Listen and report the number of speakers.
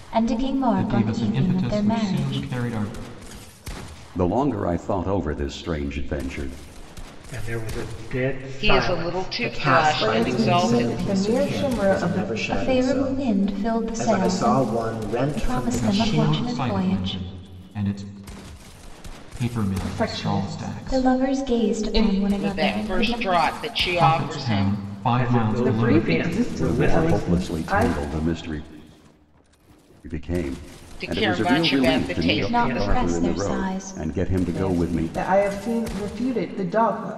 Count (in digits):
7